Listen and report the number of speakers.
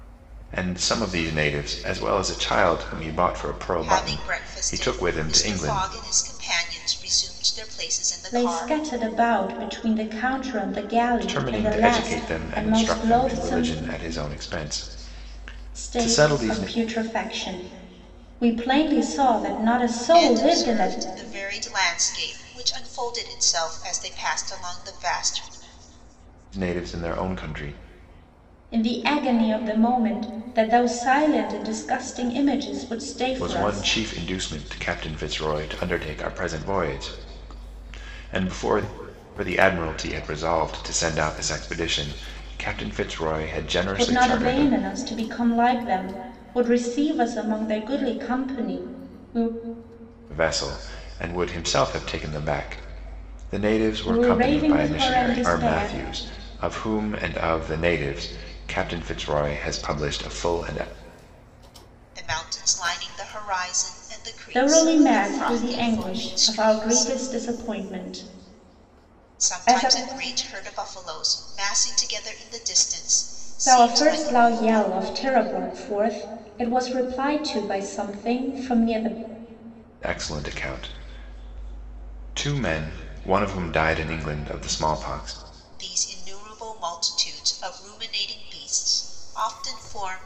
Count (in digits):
3